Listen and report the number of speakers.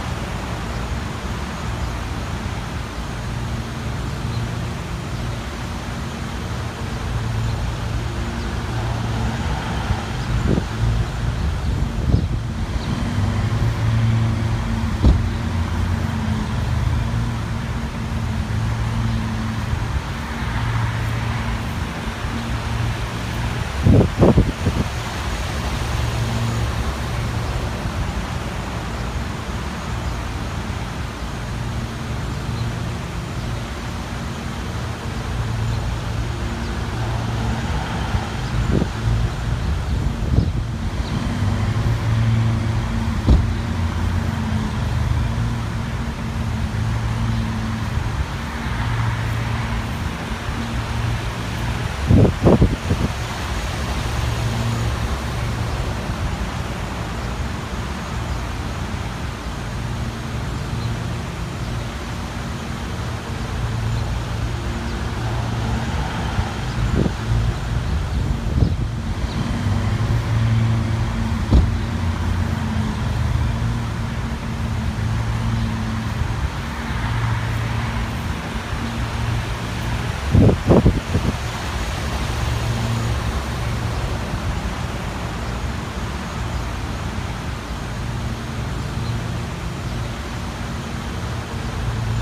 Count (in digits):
0